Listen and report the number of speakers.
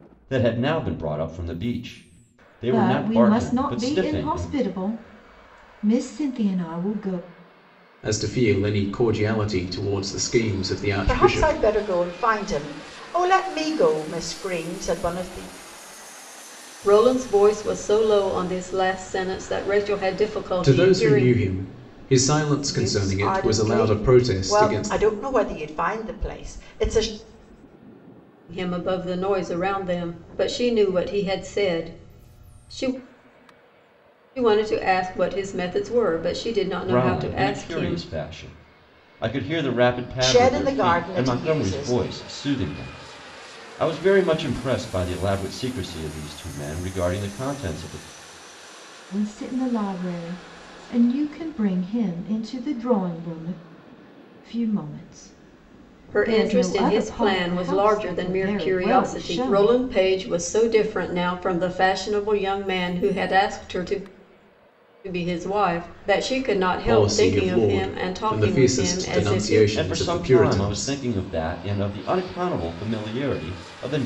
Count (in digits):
5